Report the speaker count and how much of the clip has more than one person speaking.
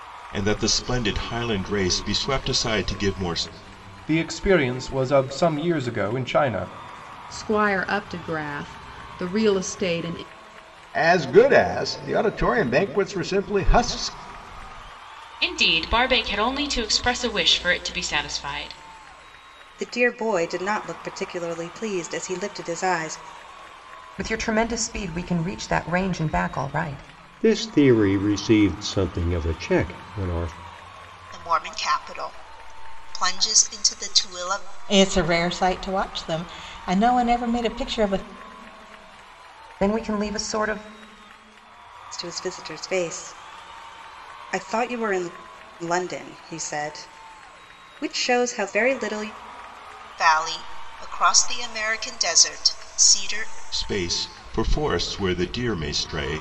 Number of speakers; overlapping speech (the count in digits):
10, no overlap